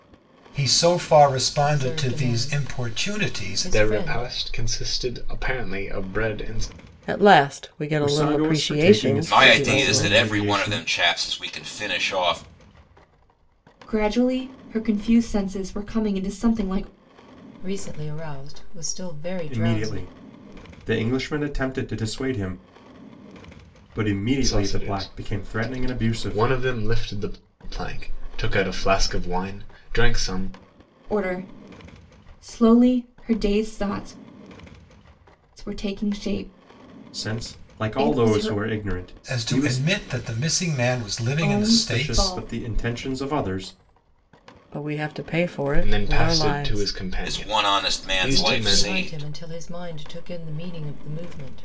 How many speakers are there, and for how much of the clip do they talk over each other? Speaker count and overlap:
7, about 28%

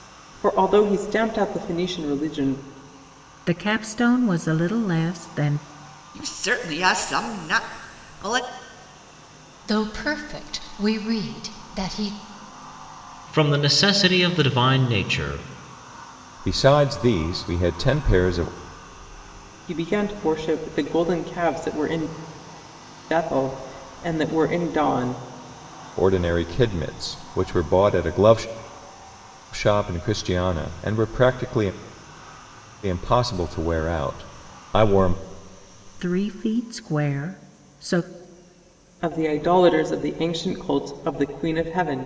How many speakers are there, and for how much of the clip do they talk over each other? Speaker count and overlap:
6, no overlap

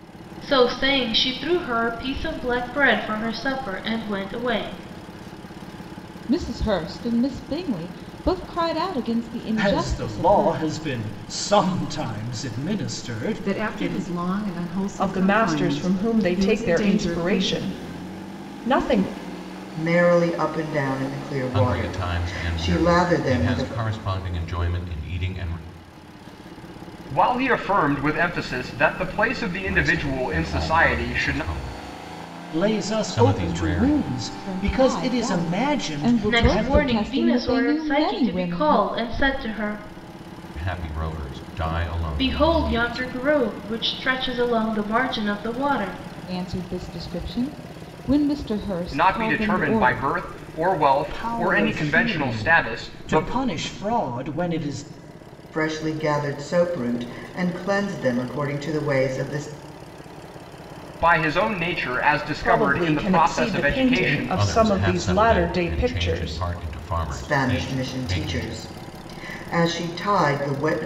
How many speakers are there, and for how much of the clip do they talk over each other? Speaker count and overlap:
8, about 34%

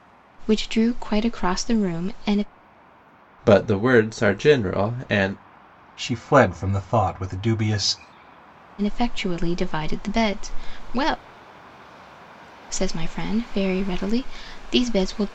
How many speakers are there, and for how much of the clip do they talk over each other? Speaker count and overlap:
3, no overlap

